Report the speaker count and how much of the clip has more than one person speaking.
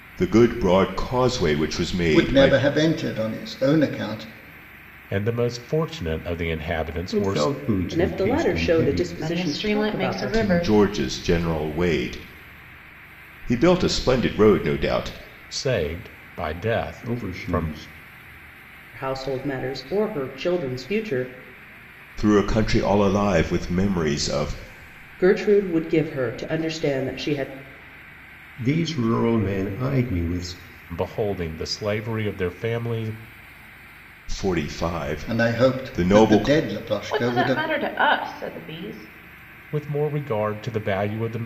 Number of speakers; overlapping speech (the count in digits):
6, about 15%